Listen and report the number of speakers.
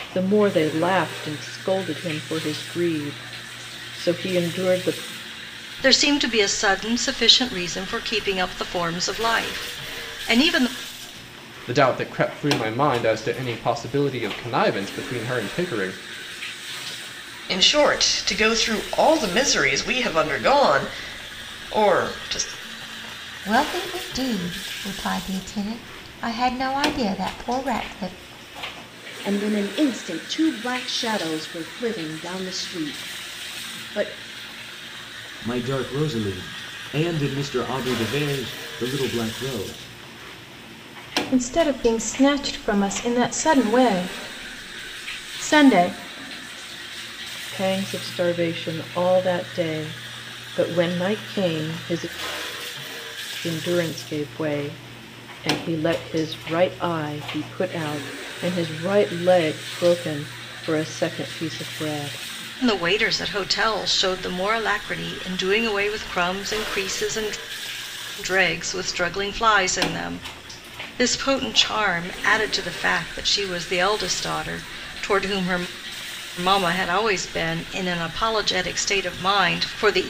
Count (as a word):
eight